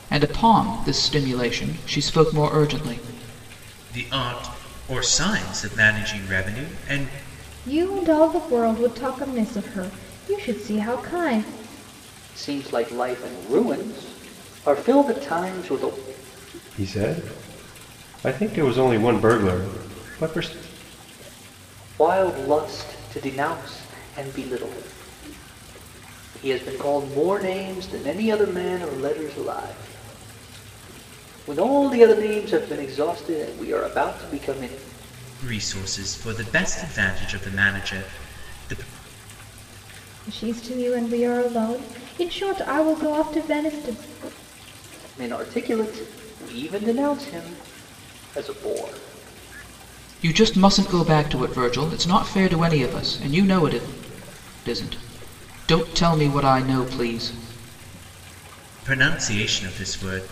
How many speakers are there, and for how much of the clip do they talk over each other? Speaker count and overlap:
5, no overlap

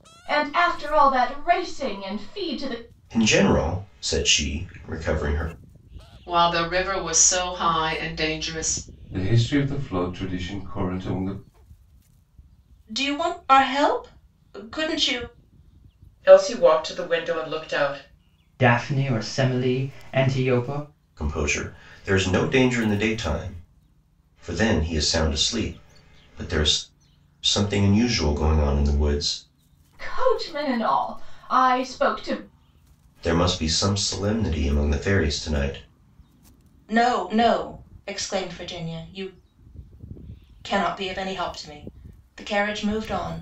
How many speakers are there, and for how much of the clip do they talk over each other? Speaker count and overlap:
7, no overlap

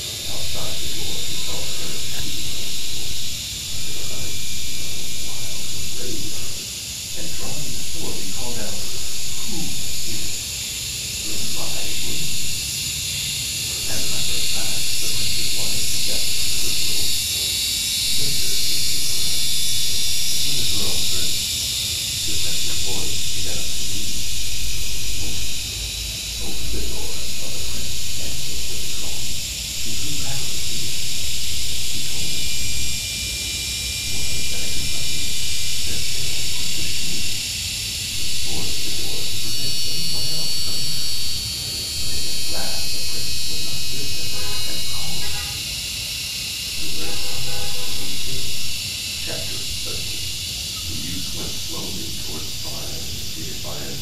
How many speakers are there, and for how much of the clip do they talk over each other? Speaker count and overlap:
1, no overlap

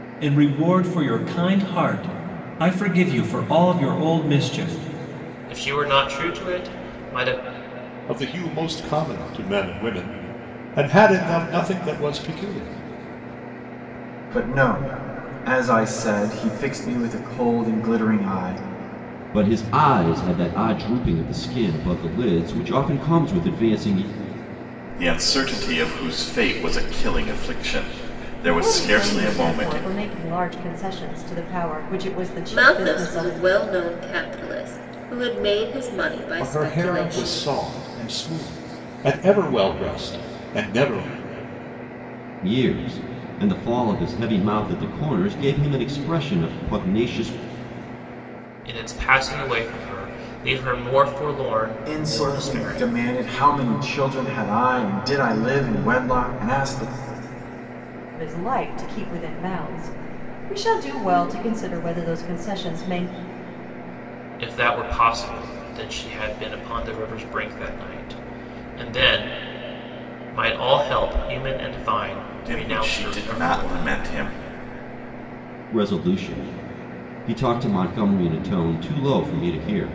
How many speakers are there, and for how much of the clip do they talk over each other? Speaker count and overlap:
8, about 7%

